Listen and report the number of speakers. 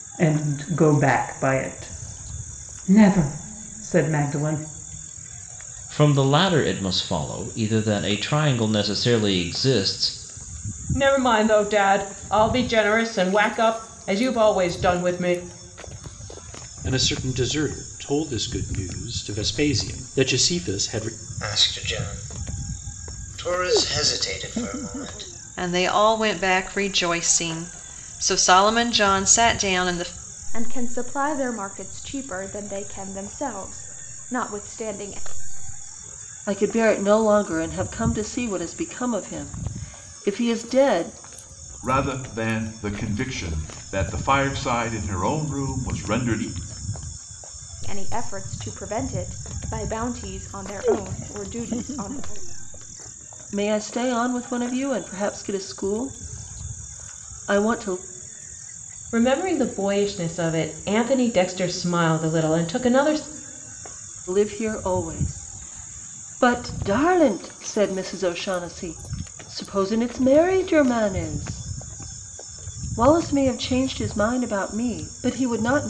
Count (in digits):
9